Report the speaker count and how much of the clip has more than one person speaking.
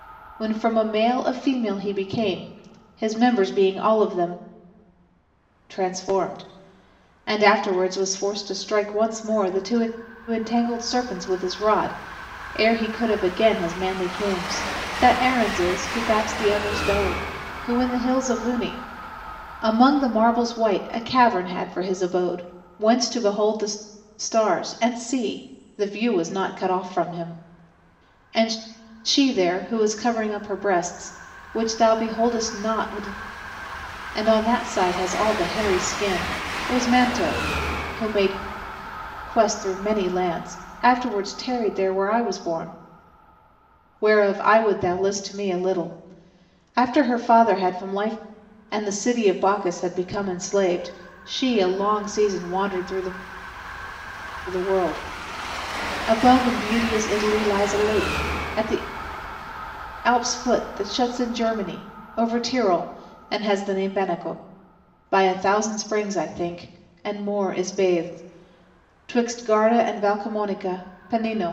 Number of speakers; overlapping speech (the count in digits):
1, no overlap